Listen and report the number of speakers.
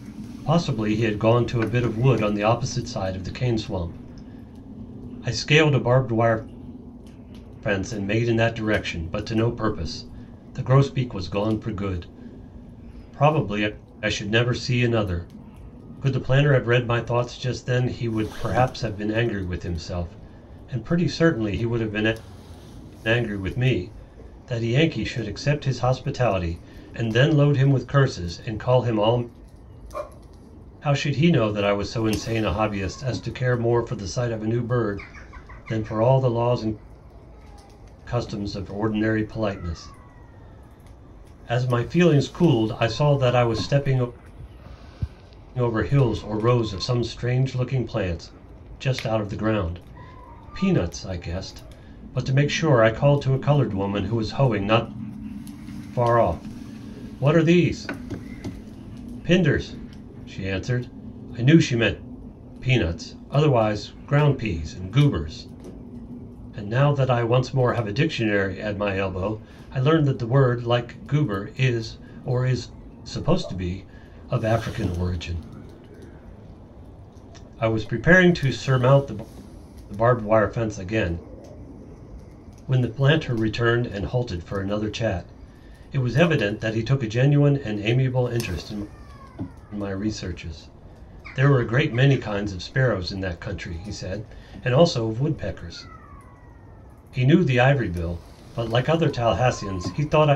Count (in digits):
1